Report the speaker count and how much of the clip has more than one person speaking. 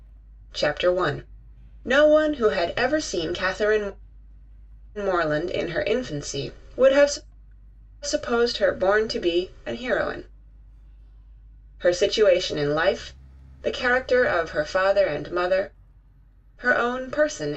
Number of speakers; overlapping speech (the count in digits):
1, no overlap